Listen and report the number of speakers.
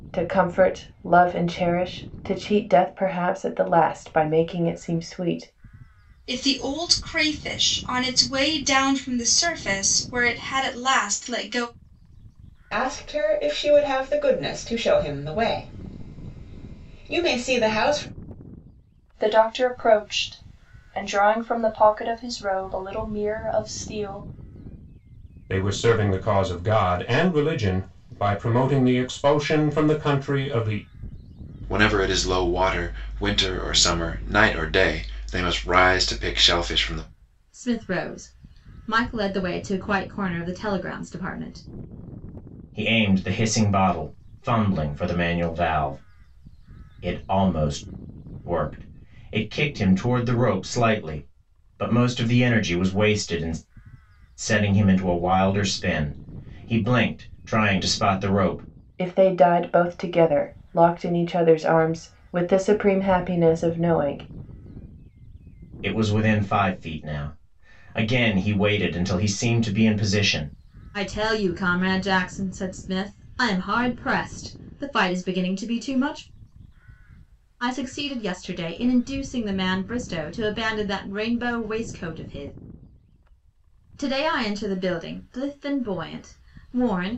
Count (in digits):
8